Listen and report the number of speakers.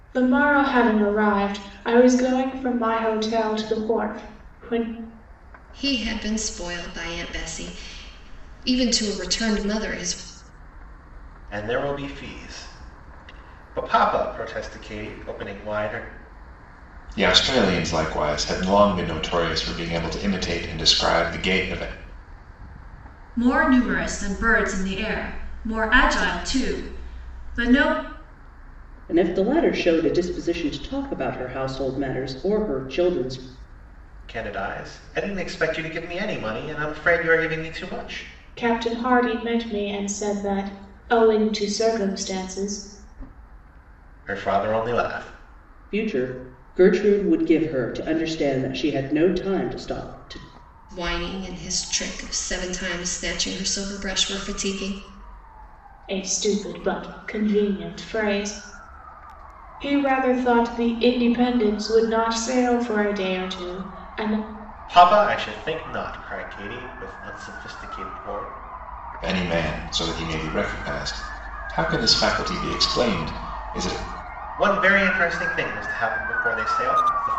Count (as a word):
six